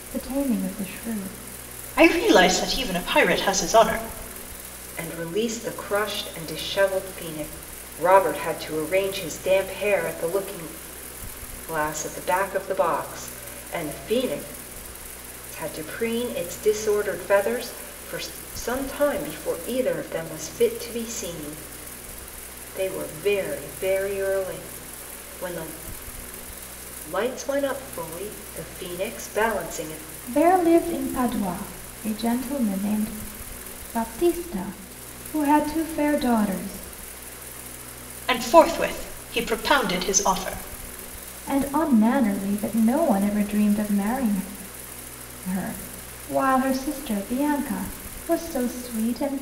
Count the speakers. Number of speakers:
3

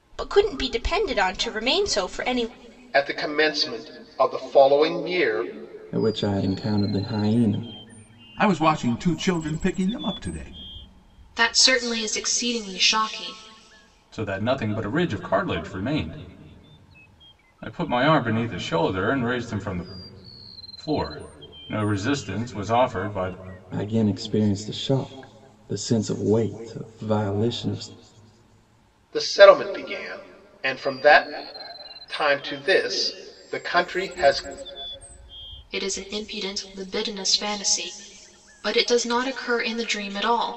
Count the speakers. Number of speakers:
6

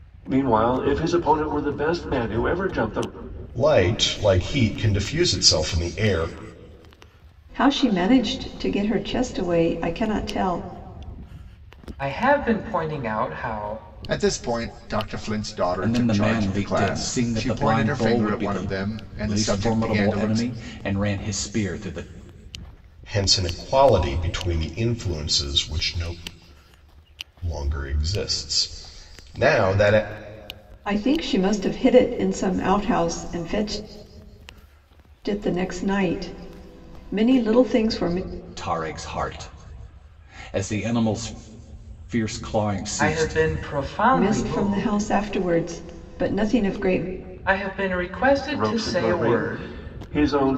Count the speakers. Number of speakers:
6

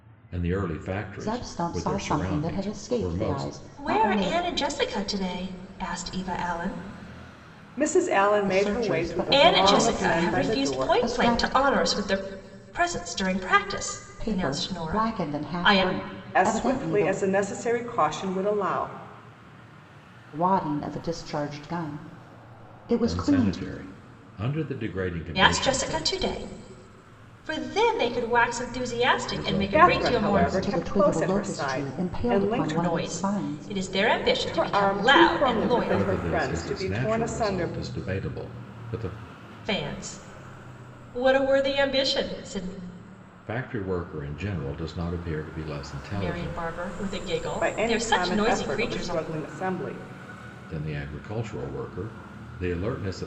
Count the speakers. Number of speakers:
4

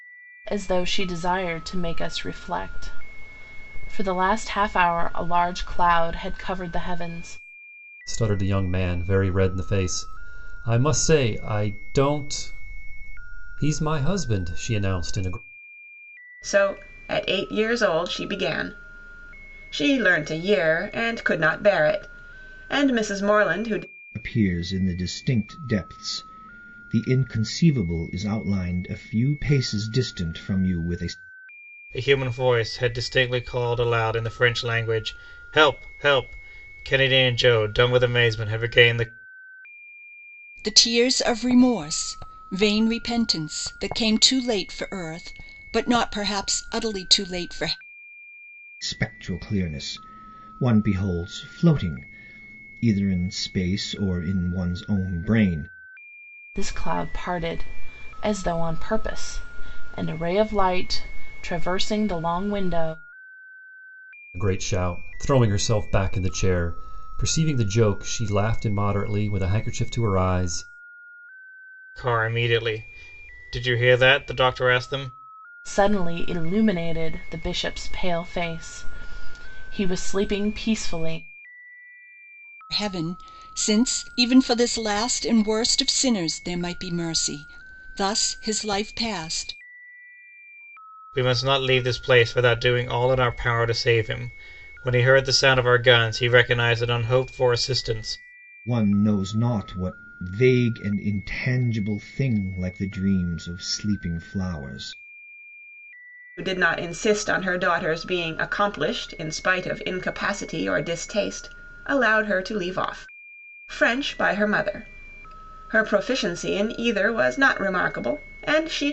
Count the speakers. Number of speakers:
6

